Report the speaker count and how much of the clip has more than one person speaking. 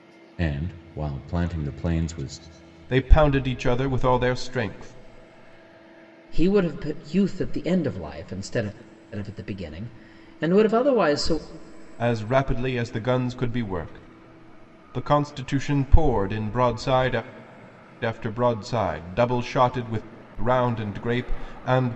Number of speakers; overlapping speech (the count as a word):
three, no overlap